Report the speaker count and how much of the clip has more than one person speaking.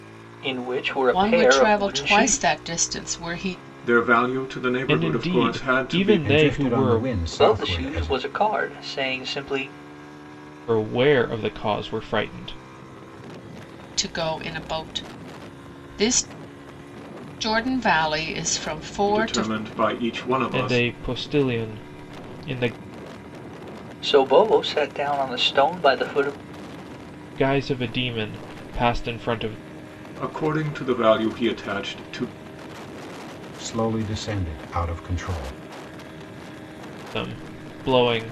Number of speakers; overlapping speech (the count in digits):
5, about 14%